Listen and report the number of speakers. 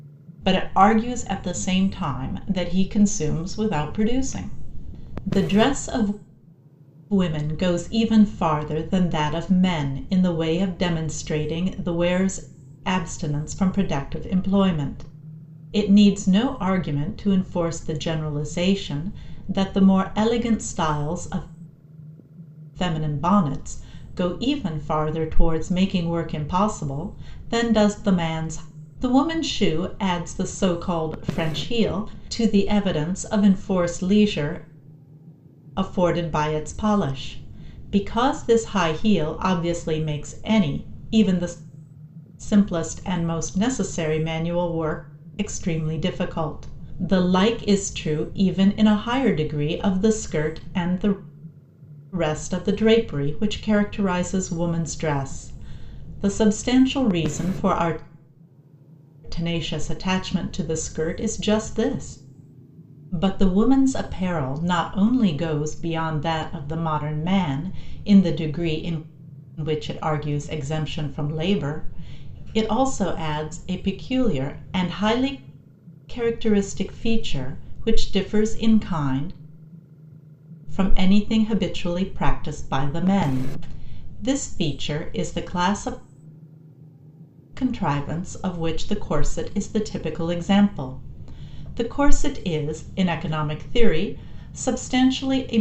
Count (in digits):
1